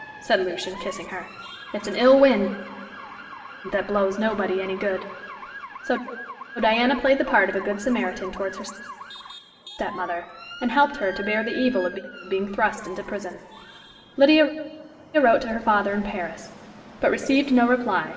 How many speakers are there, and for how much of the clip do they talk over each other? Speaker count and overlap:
1, no overlap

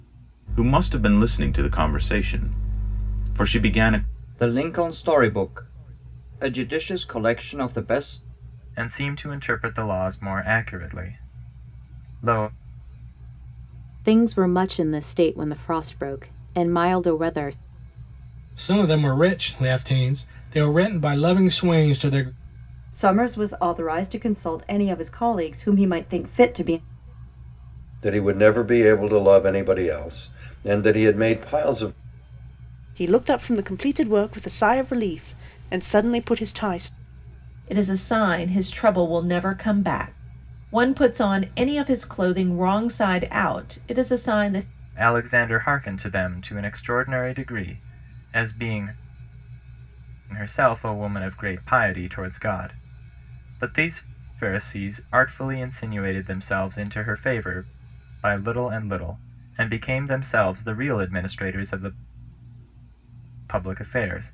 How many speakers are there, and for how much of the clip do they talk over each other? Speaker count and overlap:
9, no overlap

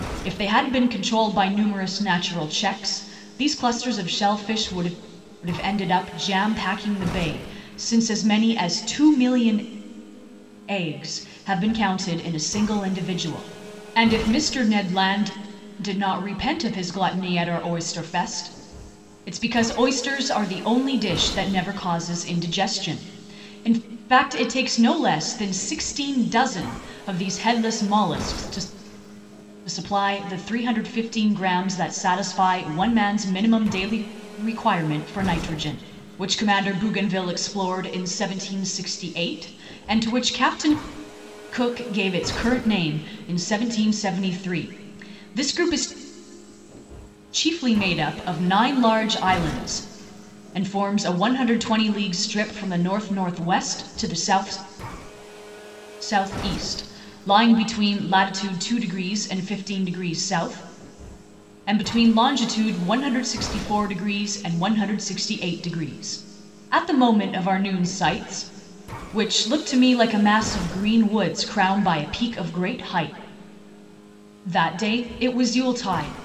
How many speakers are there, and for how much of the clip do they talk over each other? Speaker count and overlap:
1, no overlap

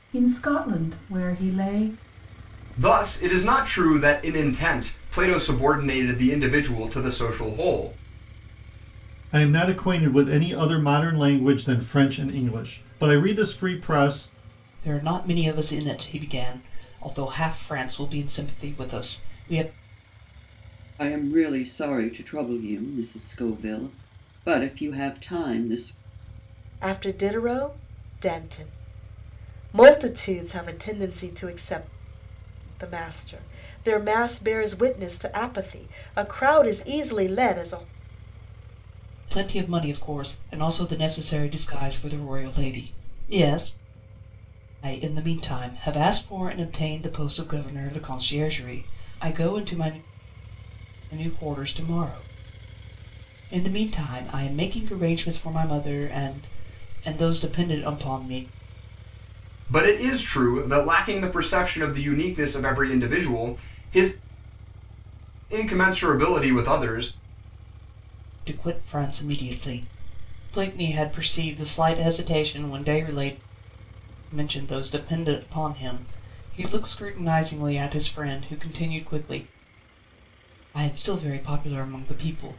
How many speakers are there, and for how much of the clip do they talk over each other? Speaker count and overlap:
6, no overlap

